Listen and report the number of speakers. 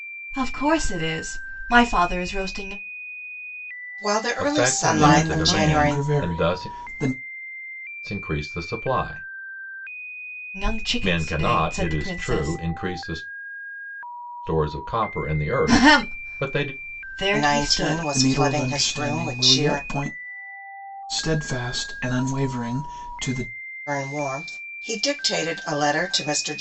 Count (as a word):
four